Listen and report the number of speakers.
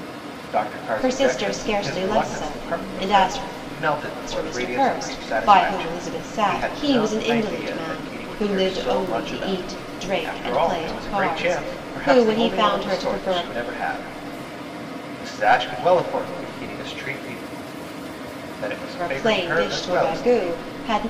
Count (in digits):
2